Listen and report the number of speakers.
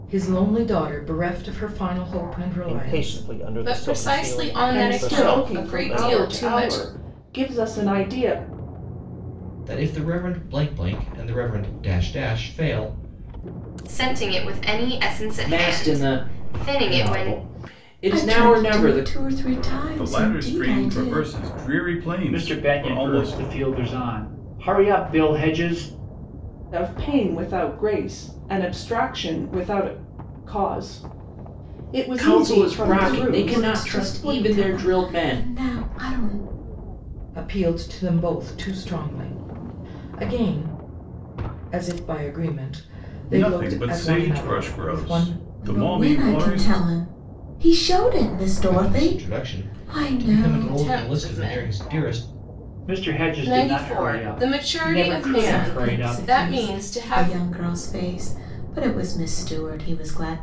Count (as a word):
ten